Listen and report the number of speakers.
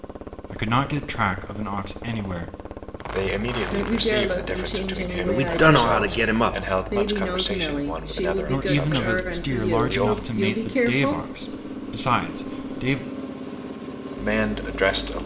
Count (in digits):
4